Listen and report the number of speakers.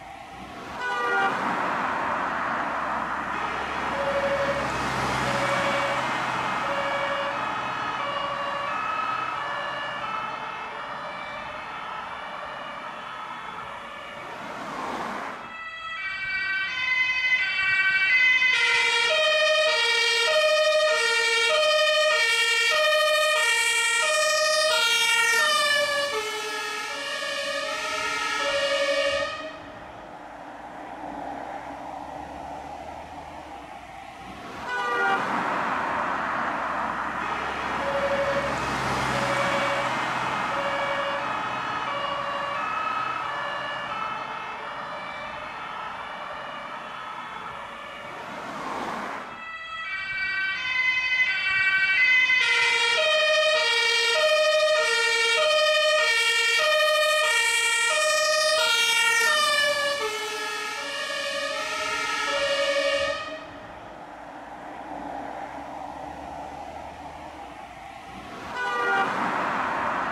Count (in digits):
0